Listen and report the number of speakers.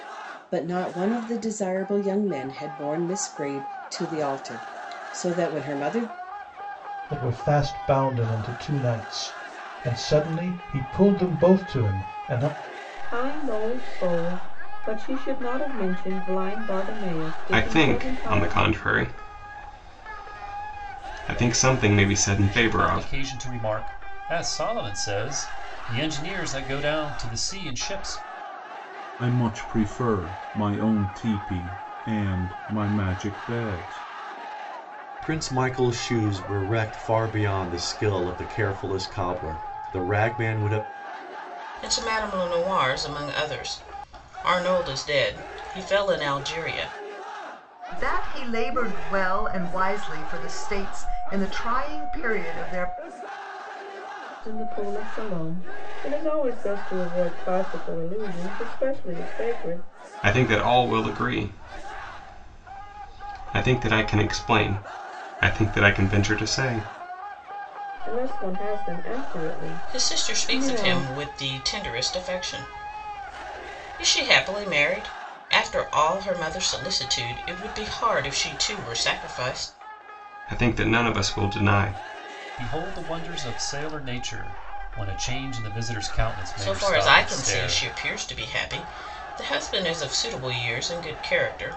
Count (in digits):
9